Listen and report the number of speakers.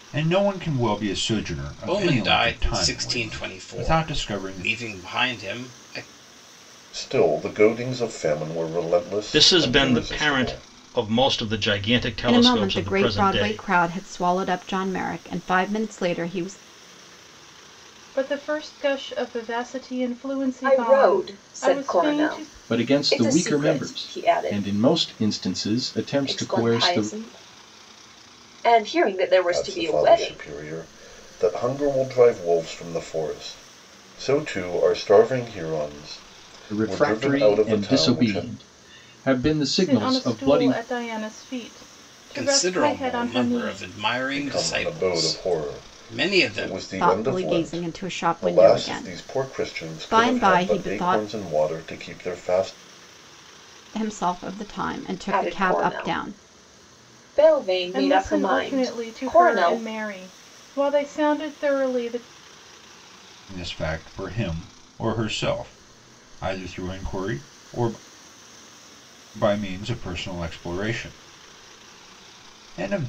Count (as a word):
eight